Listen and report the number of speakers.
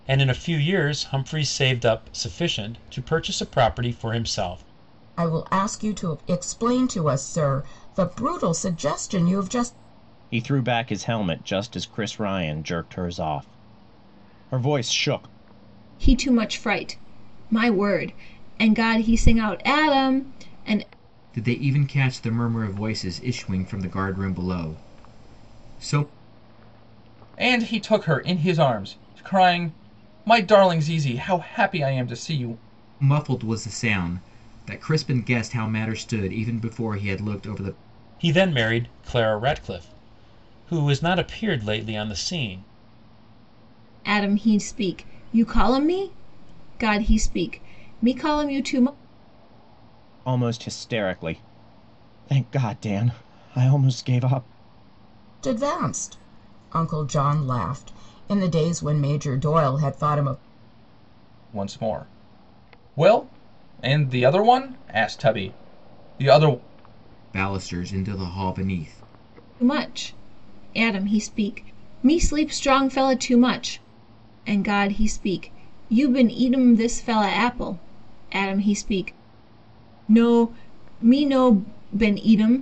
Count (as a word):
six